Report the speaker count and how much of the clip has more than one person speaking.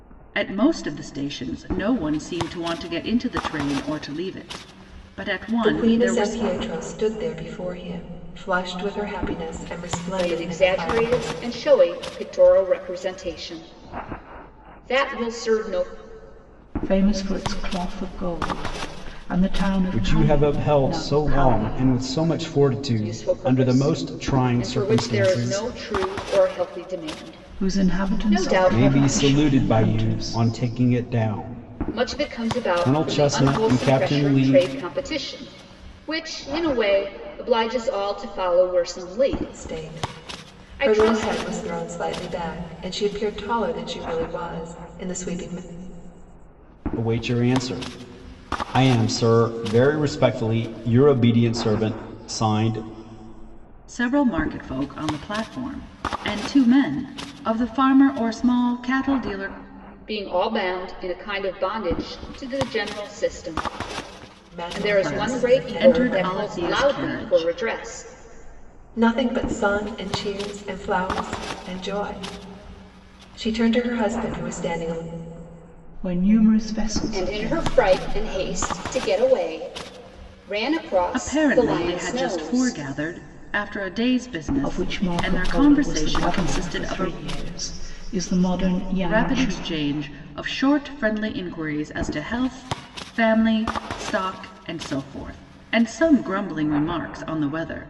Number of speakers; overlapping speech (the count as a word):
five, about 24%